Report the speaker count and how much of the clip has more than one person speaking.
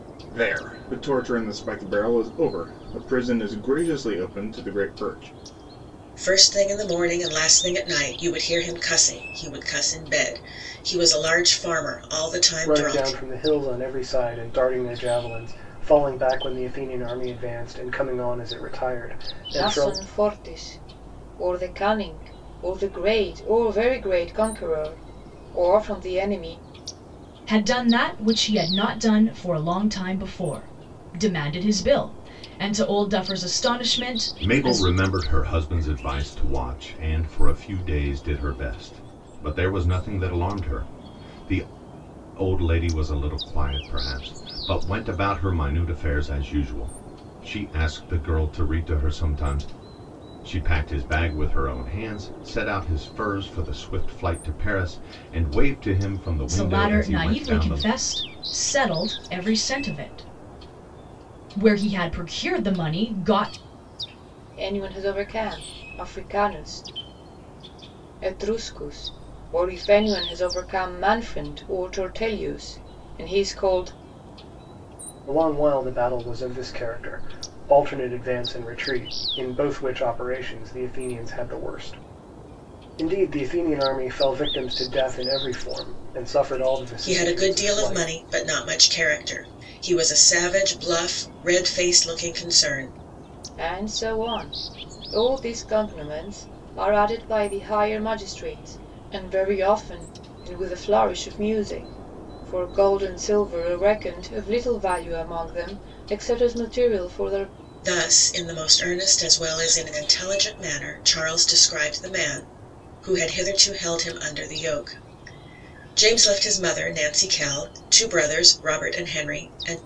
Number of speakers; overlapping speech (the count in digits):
6, about 3%